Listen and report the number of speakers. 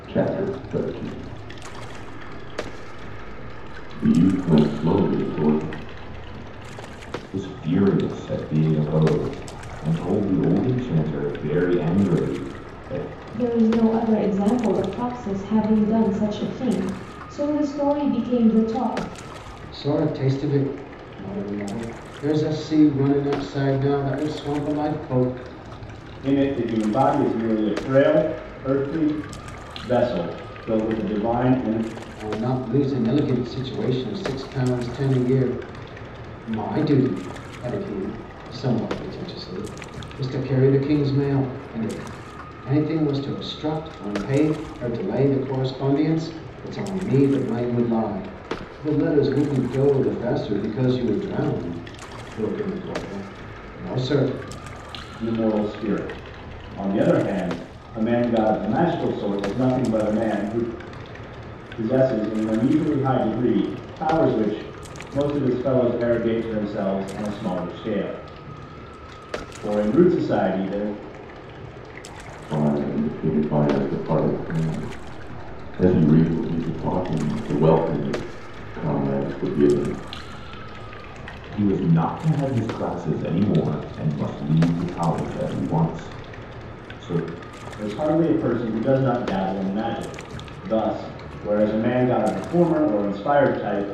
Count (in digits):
5